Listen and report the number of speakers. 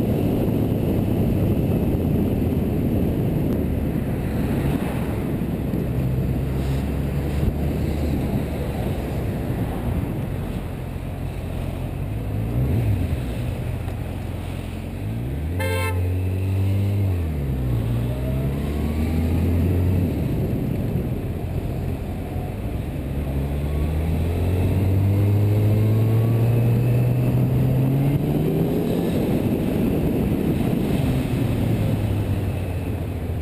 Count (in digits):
0